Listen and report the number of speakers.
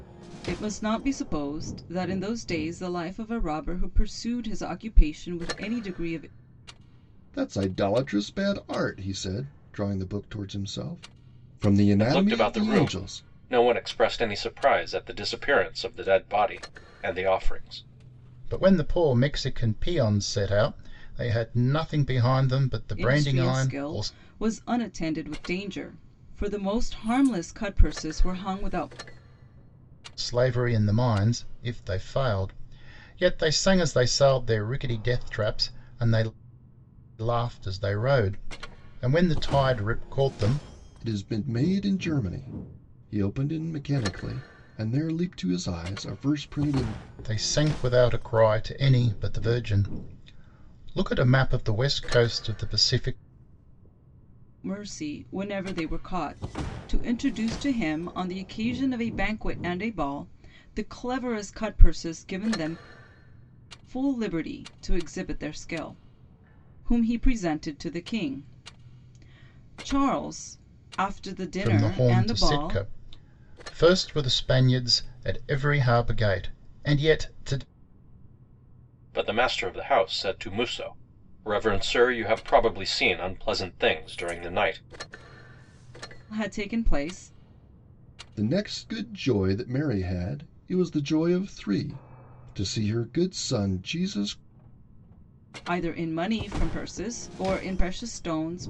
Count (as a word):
four